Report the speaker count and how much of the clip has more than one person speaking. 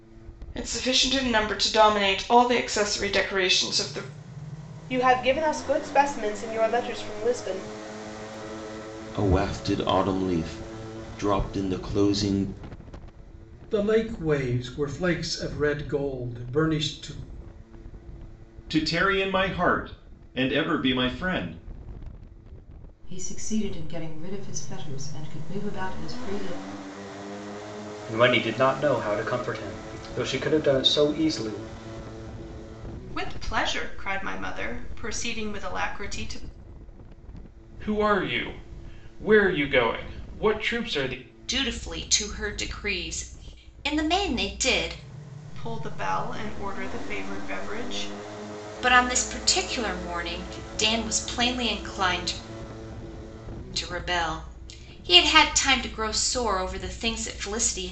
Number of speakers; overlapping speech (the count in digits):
10, no overlap